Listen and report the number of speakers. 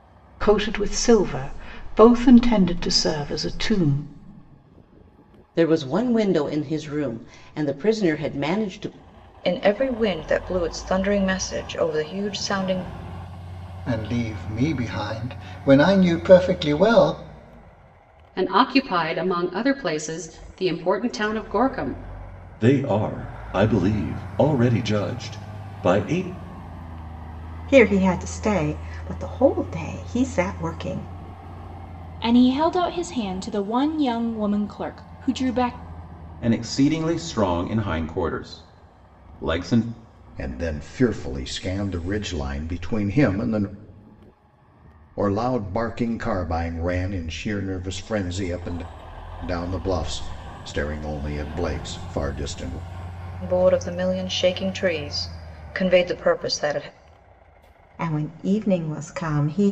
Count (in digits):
10